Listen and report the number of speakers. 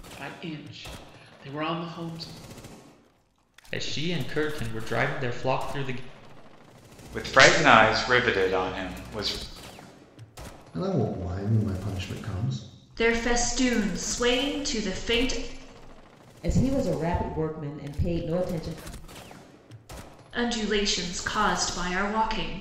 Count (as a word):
six